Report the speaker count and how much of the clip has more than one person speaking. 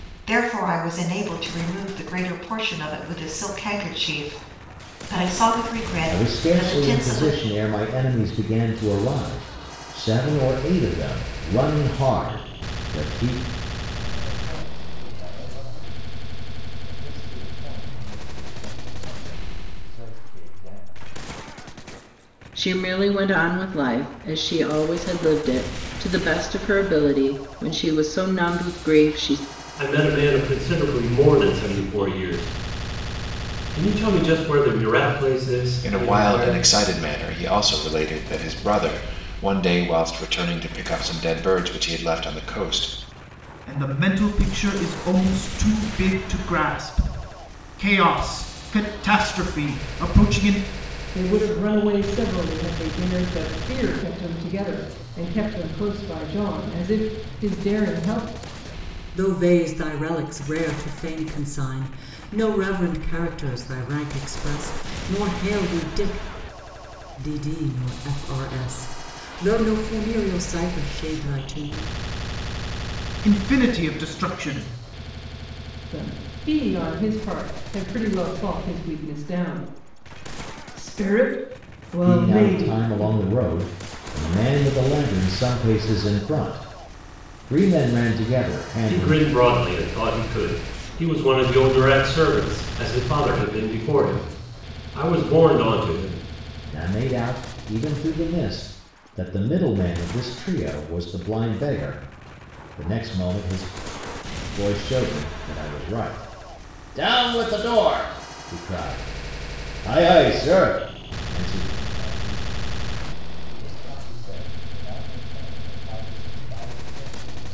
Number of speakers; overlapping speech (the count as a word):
nine, about 4%